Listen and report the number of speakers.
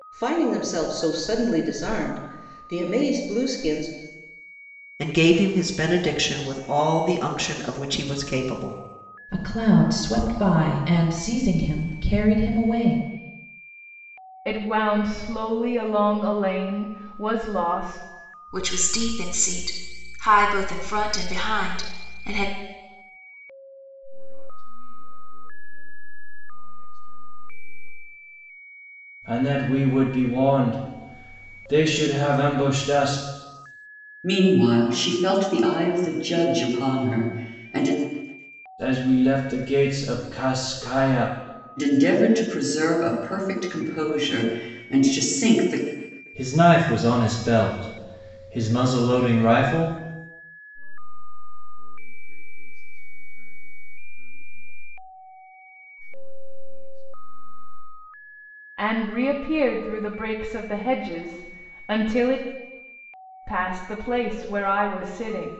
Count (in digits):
8